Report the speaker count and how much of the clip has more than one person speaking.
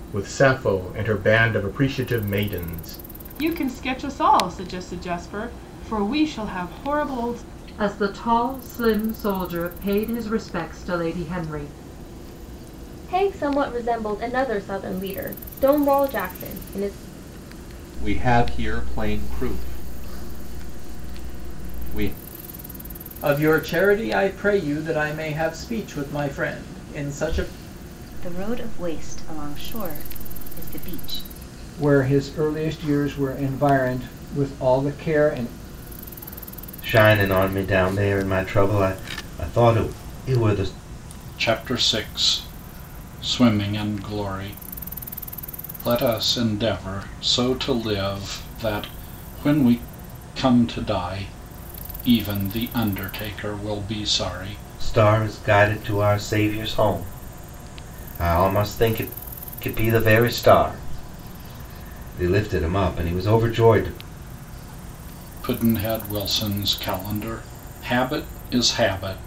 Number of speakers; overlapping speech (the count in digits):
10, no overlap